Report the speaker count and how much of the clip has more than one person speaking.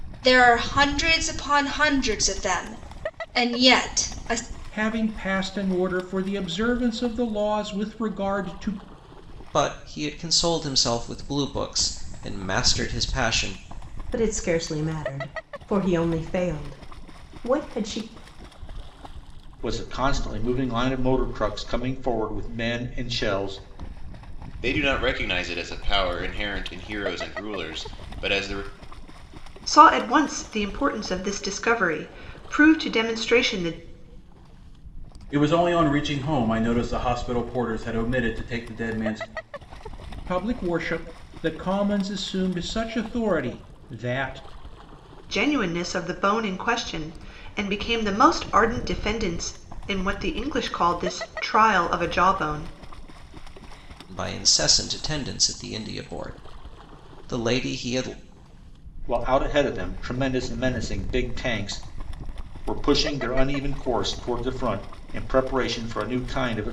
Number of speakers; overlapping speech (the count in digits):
8, no overlap